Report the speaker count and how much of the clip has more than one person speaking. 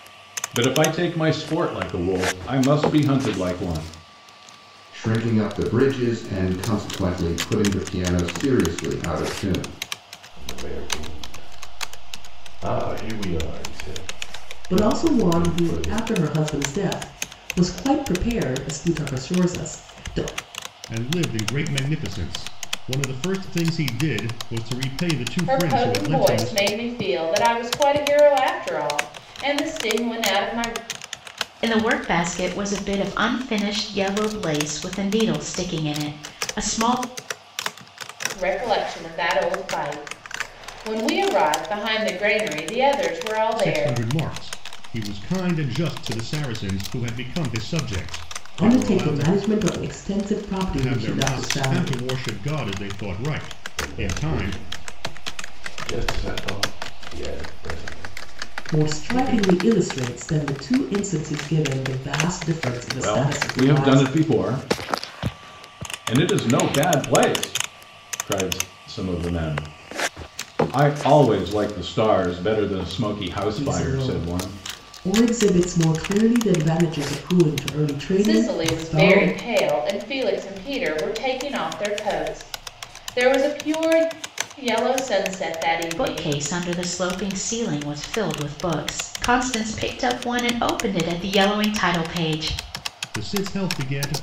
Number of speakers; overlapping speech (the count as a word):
seven, about 11%